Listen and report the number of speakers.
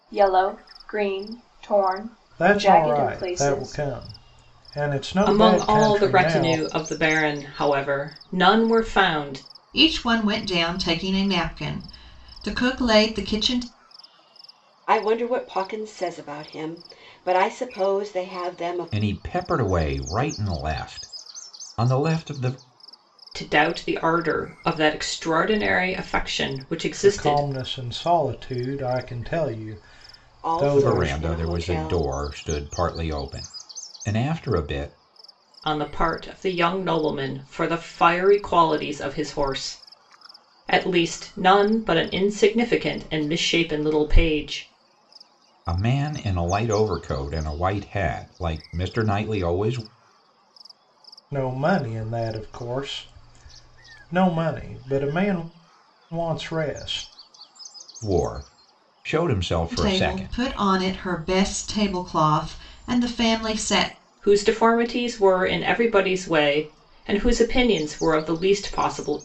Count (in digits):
6